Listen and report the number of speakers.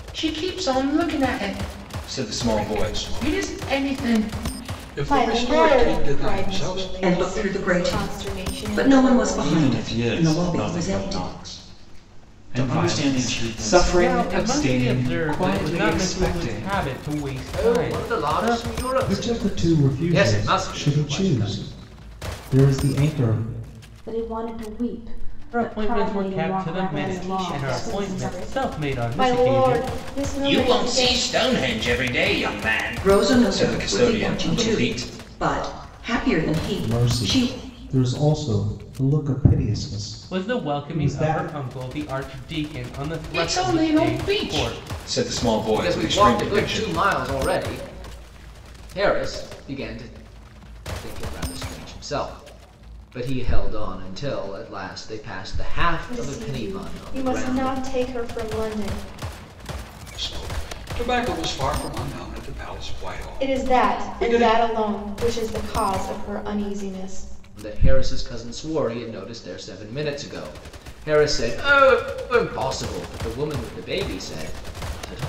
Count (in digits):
10